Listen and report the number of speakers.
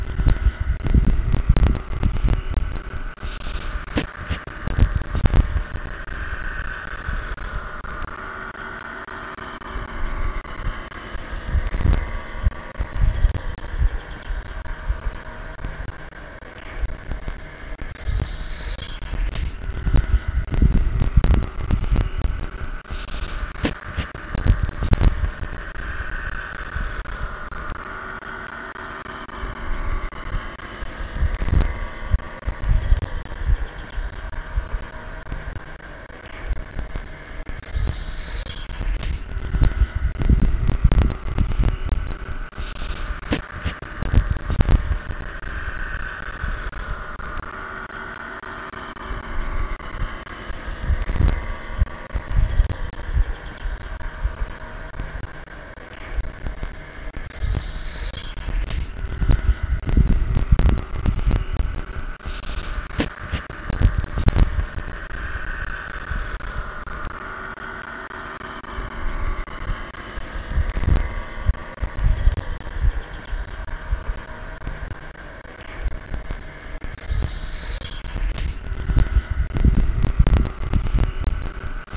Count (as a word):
zero